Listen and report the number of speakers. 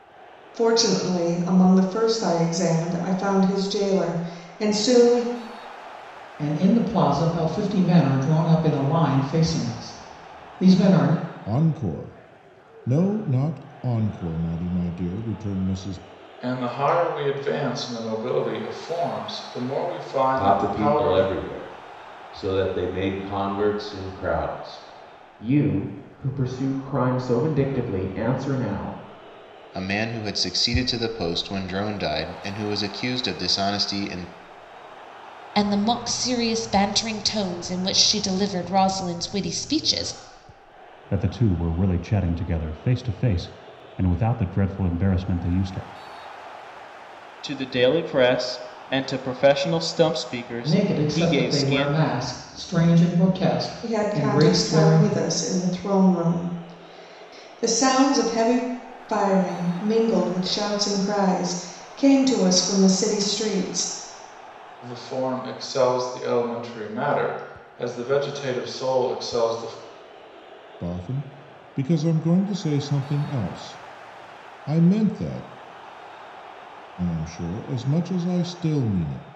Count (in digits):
10